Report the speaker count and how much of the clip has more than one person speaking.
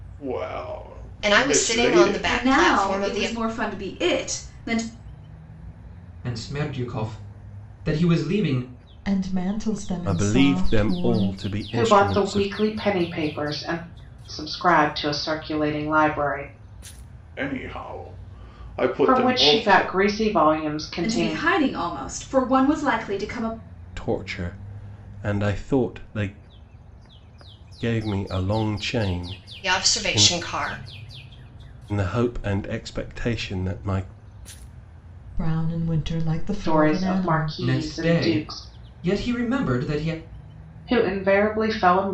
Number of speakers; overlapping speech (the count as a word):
seven, about 20%